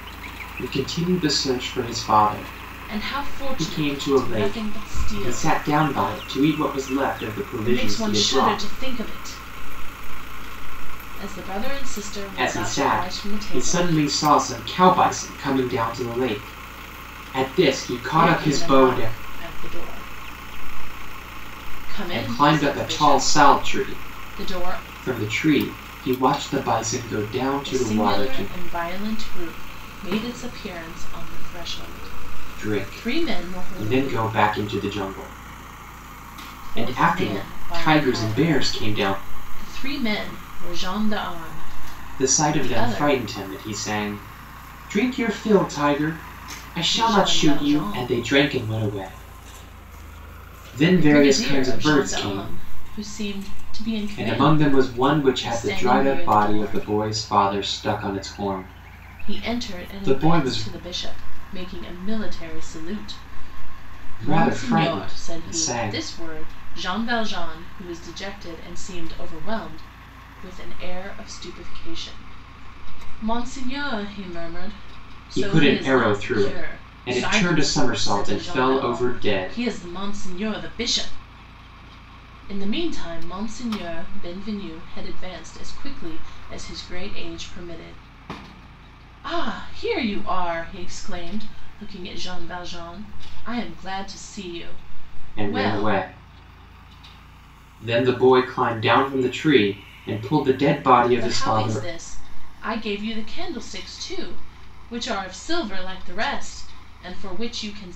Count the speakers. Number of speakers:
two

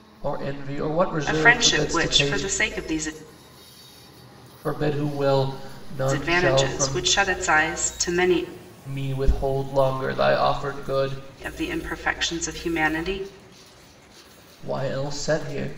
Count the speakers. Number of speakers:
two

